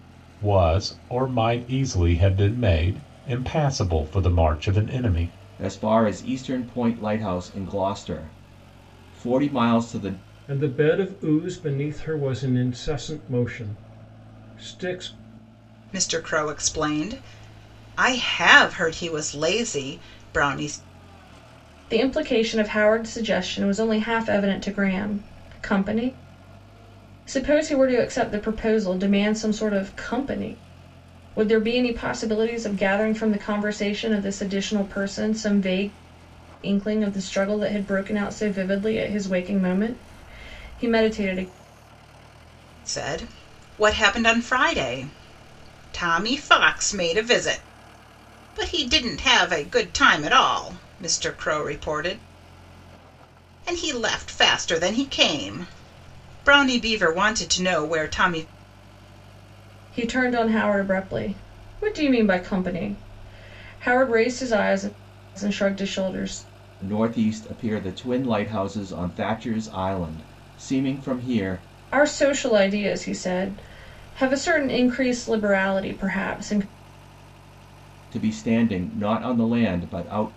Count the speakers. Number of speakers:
five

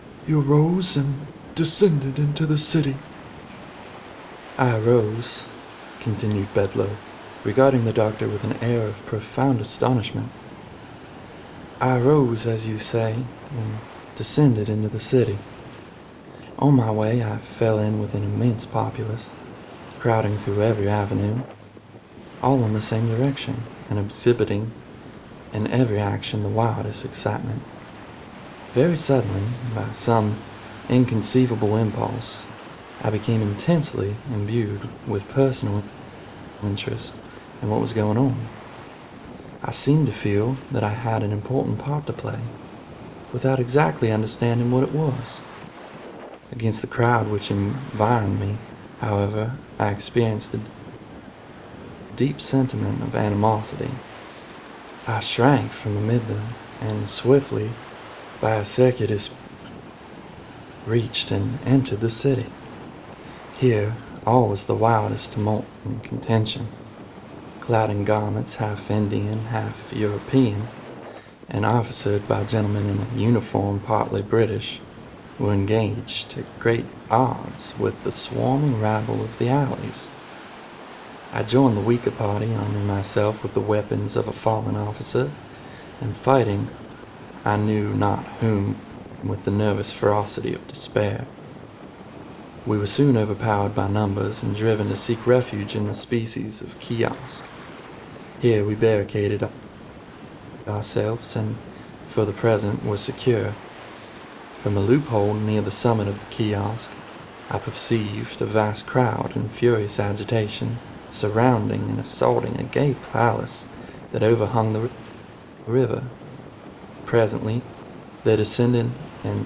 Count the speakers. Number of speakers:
one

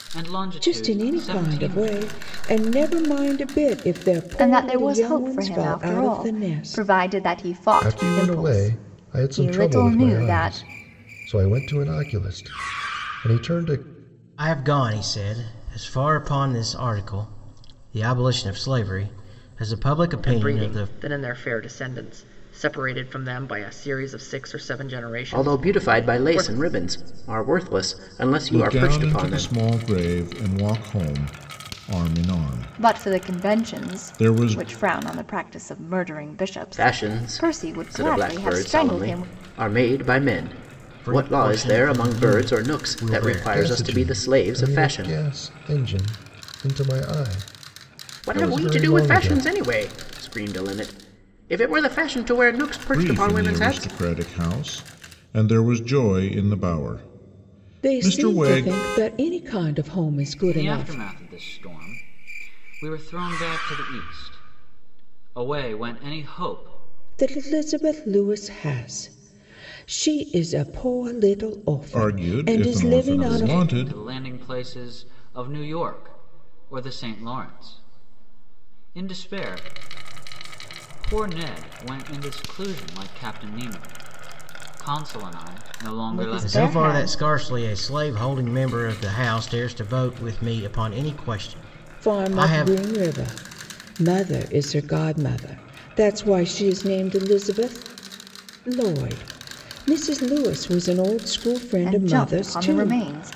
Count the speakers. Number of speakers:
eight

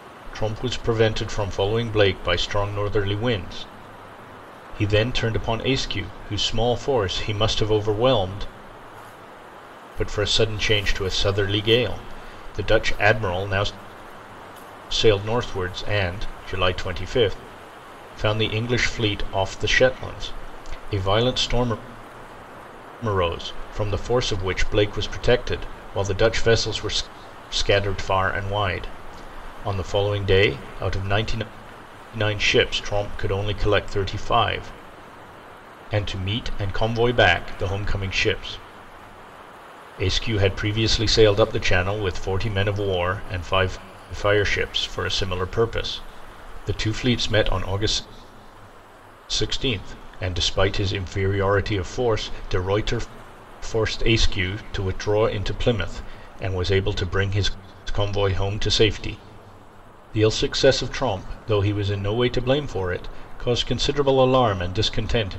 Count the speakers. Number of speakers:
one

